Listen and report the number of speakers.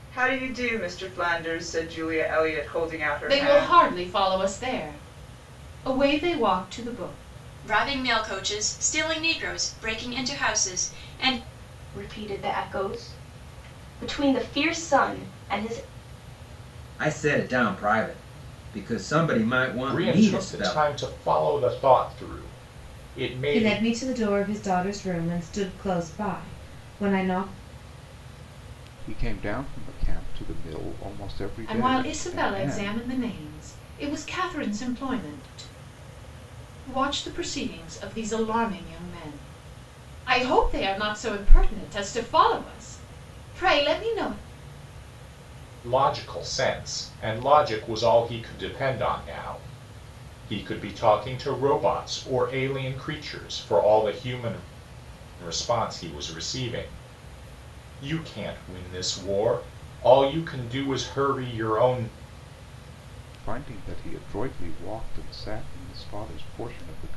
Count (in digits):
8